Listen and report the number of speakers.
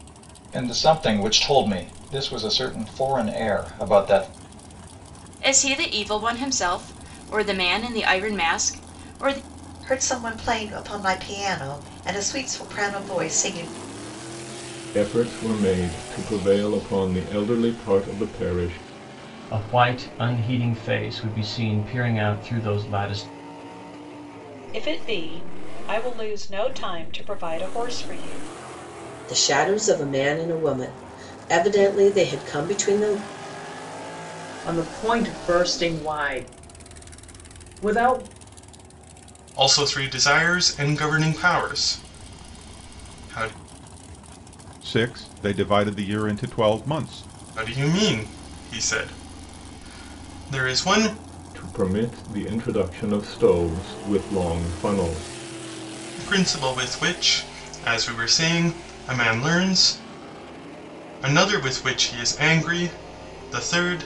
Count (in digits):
10